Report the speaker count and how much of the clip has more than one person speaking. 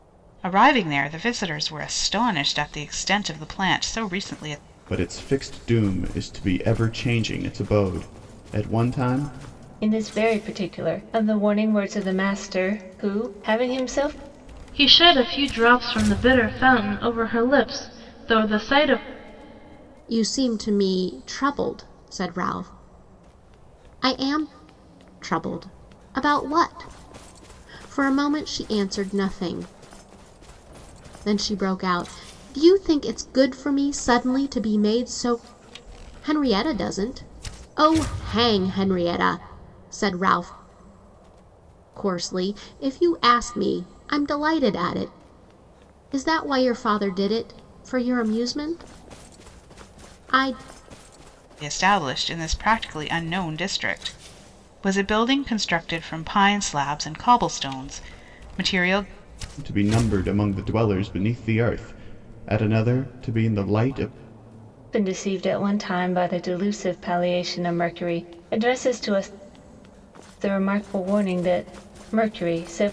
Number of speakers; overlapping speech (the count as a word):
five, no overlap